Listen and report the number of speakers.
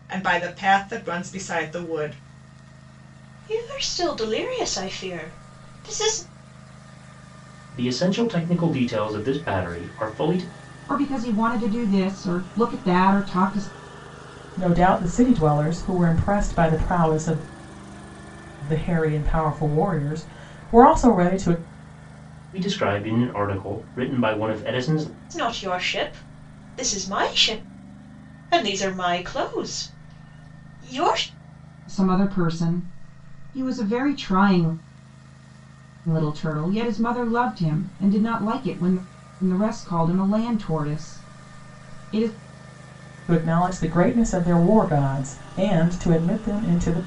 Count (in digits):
5